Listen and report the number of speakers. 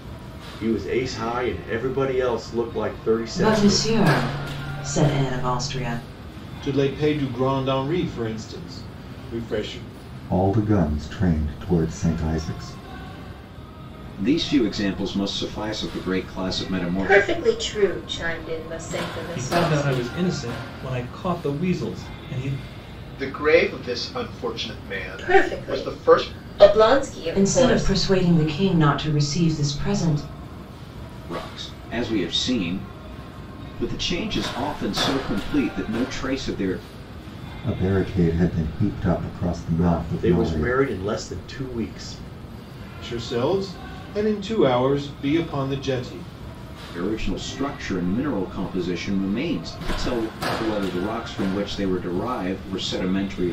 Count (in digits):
8